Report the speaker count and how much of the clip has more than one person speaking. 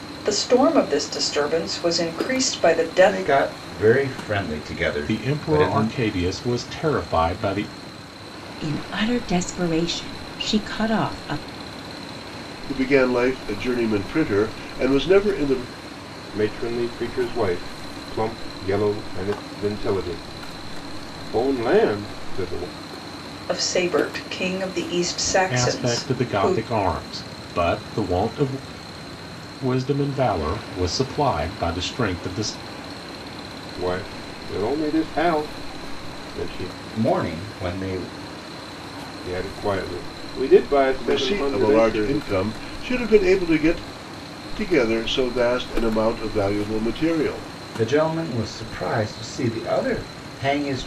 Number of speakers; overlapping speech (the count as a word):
six, about 7%